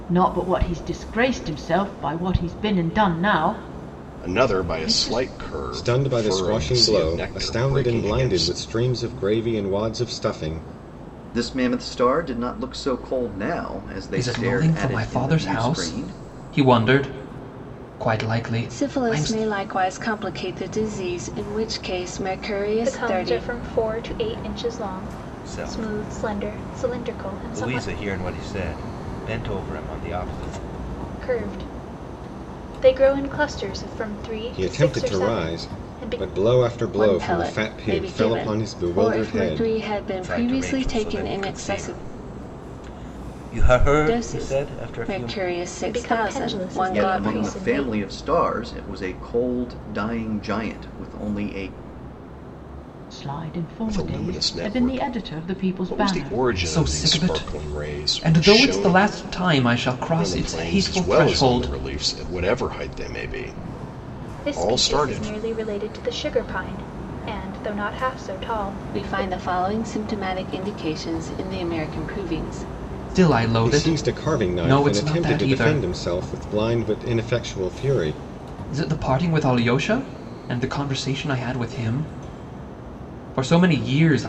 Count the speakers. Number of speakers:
8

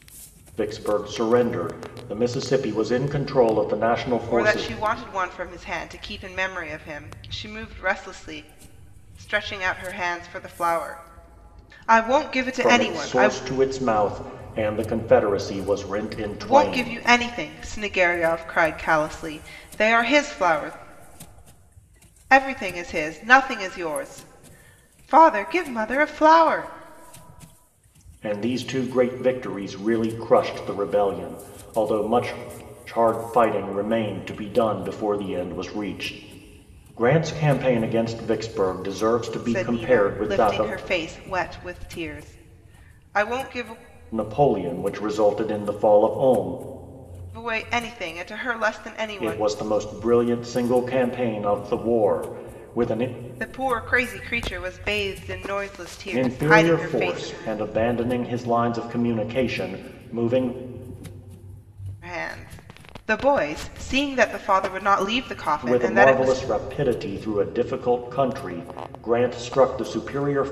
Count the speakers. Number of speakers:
2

